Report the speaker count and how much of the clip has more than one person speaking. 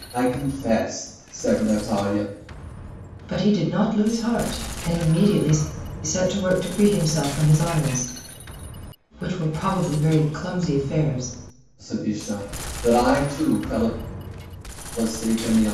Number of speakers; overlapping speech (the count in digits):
2, no overlap